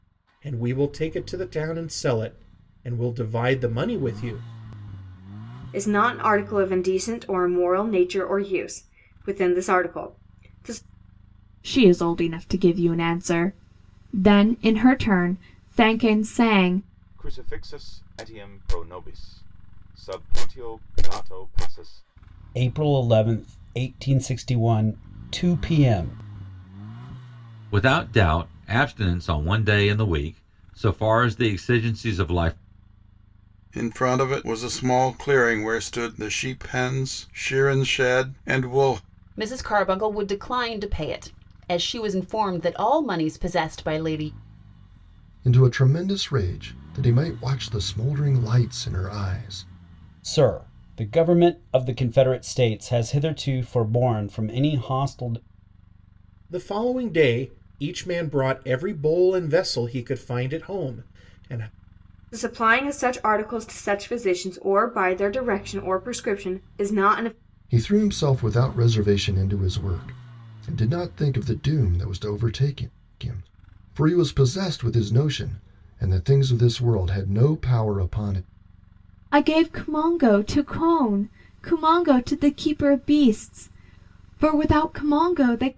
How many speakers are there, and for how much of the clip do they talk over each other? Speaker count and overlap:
nine, no overlap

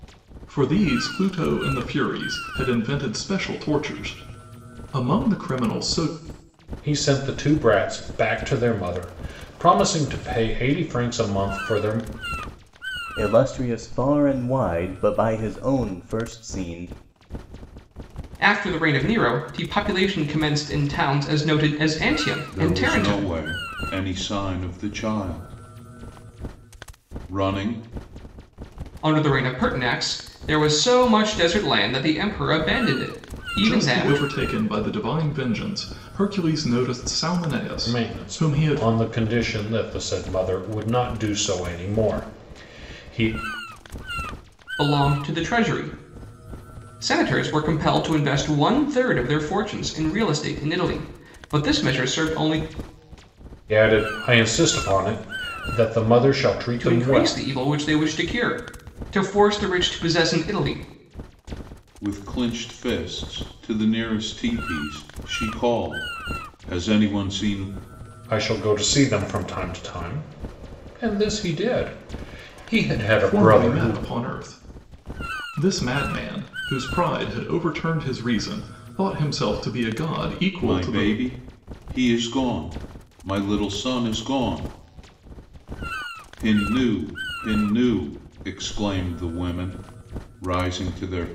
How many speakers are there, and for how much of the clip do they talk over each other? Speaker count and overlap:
five, about 5%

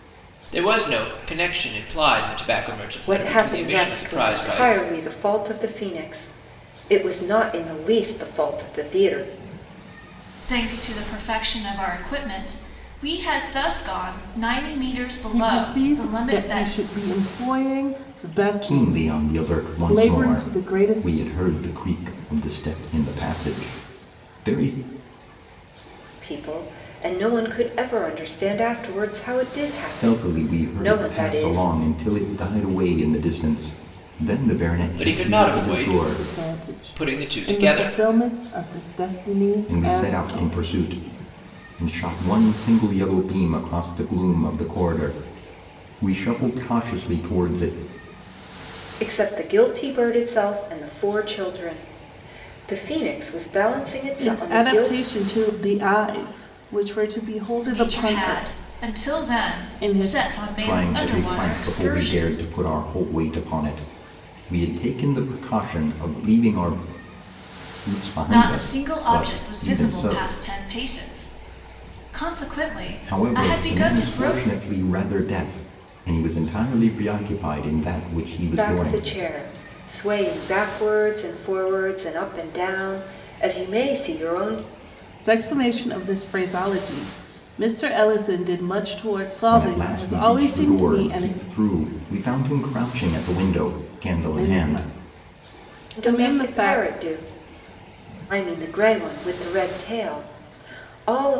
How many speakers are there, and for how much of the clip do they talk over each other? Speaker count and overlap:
five, about 24%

